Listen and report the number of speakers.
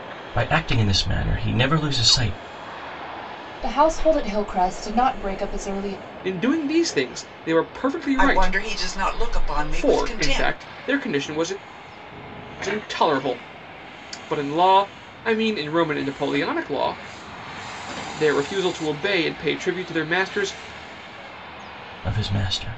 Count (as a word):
four